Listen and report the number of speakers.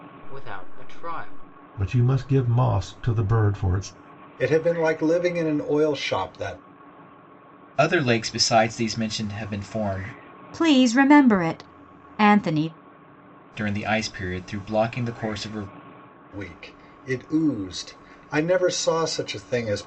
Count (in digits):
5